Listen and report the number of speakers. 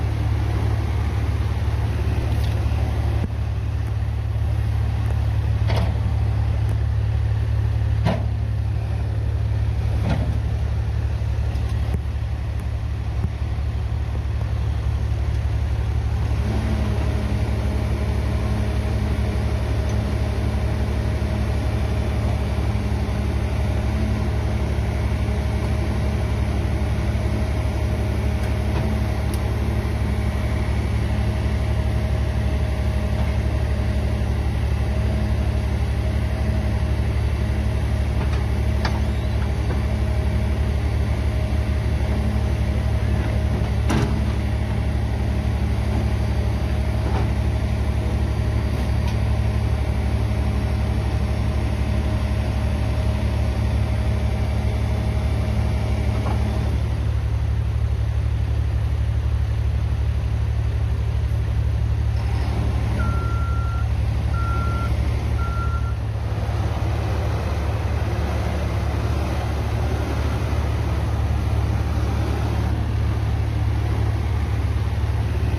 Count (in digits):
0